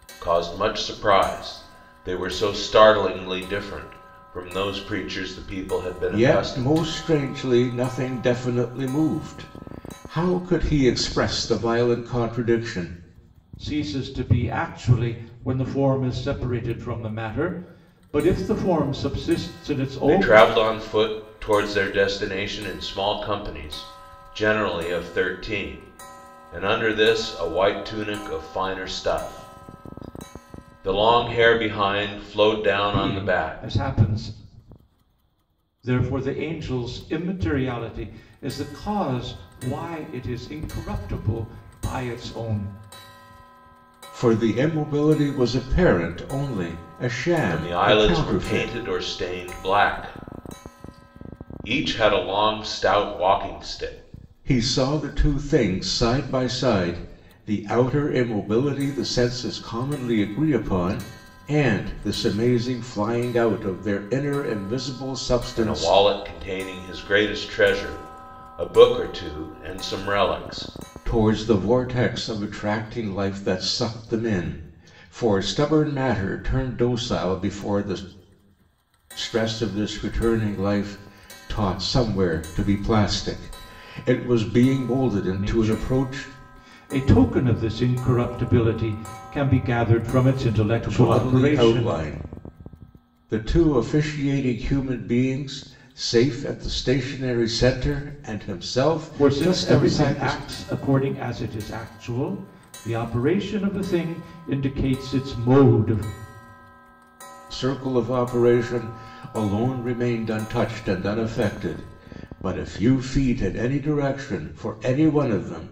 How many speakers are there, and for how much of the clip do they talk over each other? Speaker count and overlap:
three, about 6%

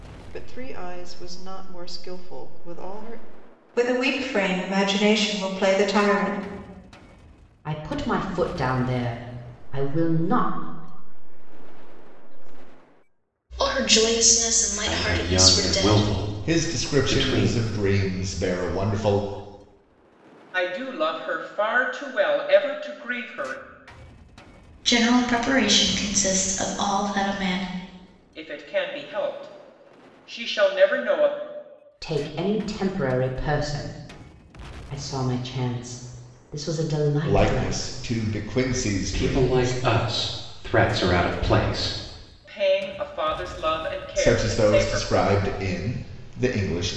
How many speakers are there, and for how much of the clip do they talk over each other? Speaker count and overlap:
nine, about 12%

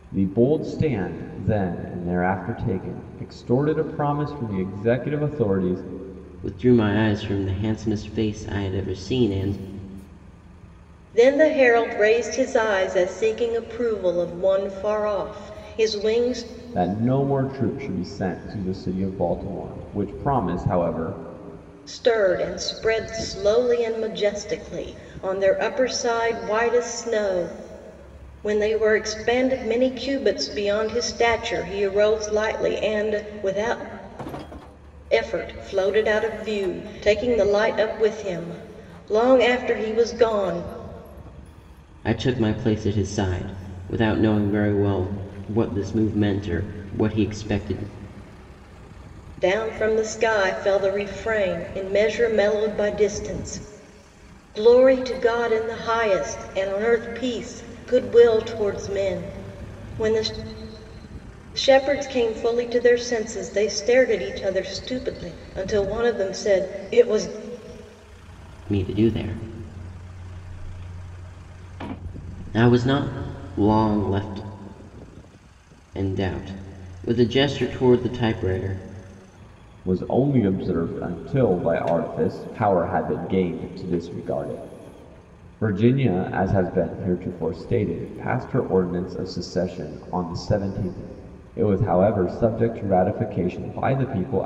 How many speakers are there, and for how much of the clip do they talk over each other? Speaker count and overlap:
three, no overlap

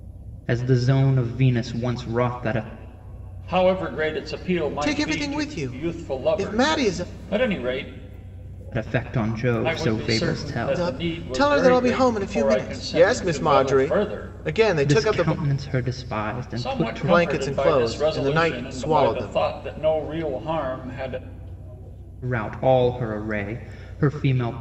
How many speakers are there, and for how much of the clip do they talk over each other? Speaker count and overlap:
three, about 41%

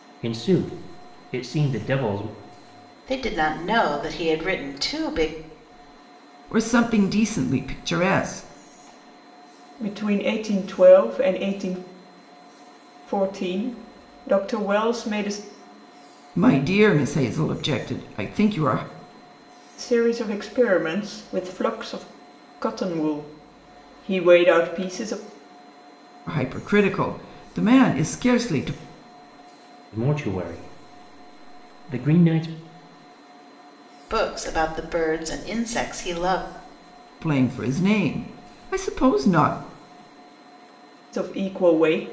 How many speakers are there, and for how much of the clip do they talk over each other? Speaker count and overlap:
four, no overlap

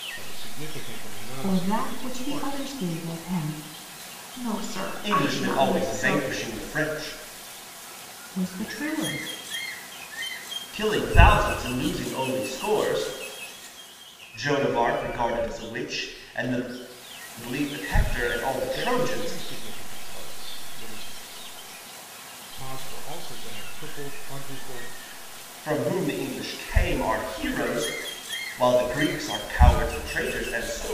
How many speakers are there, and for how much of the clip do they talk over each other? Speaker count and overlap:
four, about 10%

